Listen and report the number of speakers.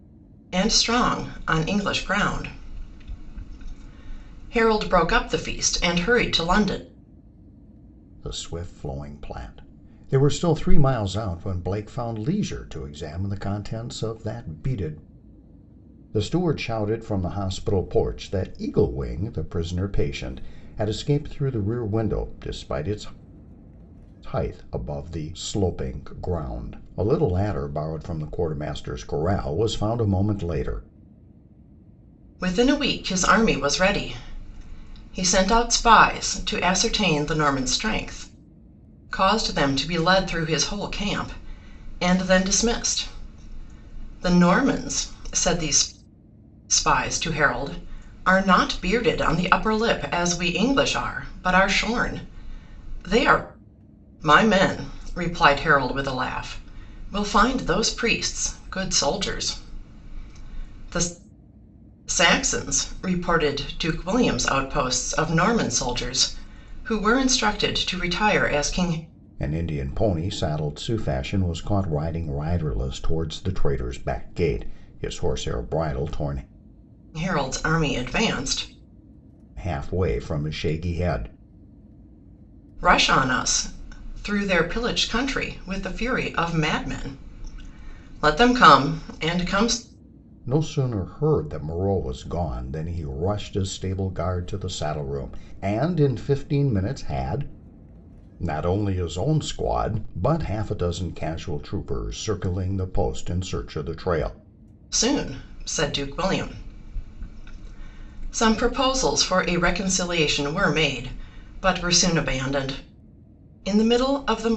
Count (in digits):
2